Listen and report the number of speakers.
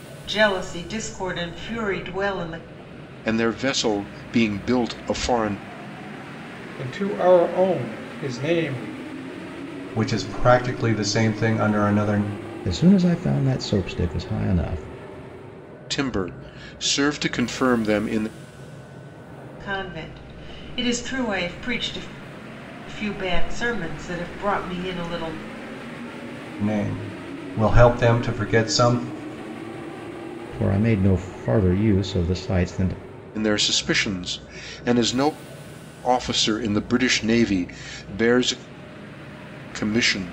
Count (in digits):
5